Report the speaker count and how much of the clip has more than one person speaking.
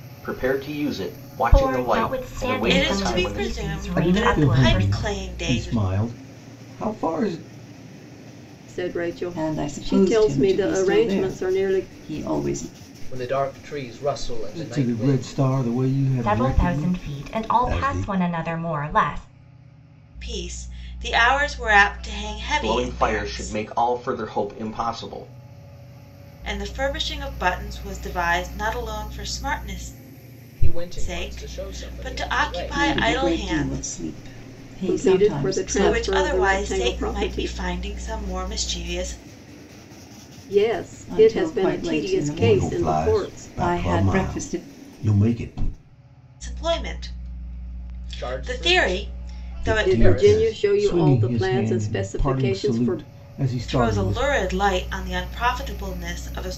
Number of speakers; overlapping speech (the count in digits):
7, about 45%